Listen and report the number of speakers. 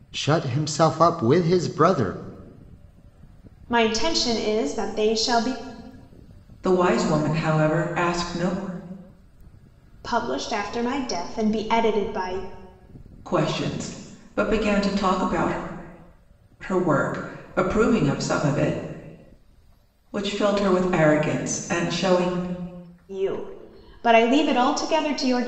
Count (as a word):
three